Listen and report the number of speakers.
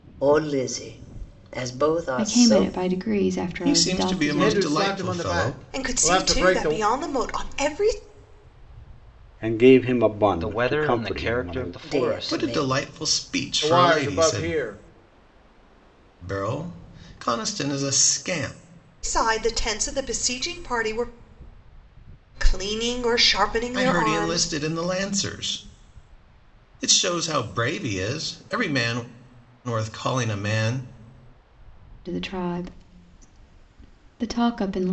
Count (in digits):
7